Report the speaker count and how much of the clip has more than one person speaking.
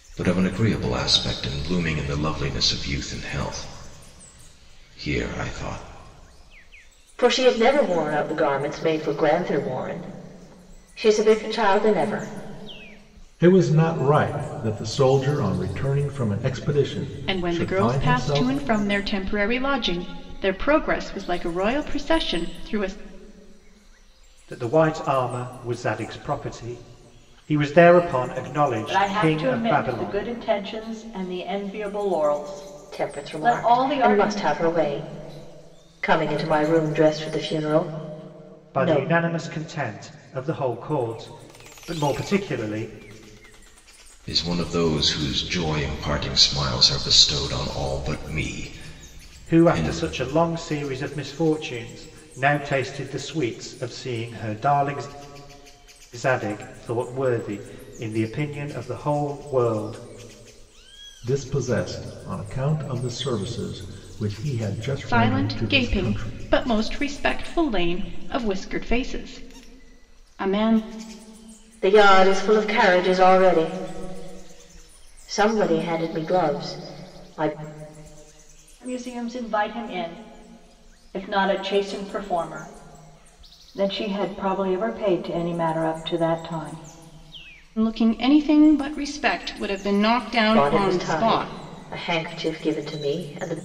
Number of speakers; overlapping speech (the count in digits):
6, about 8%